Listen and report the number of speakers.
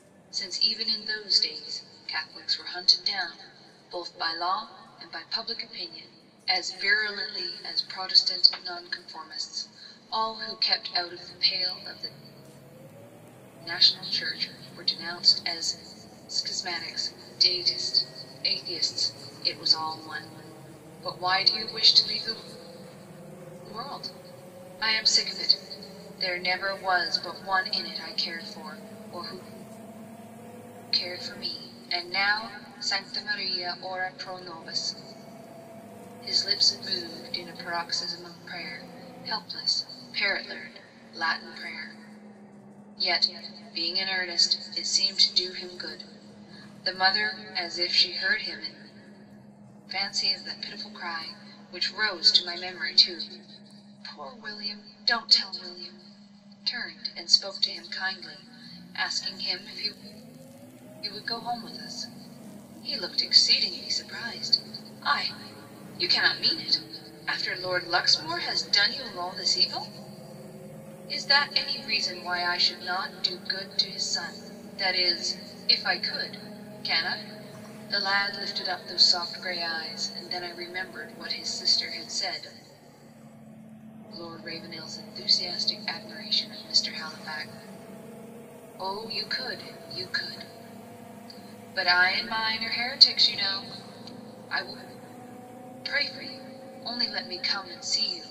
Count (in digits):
1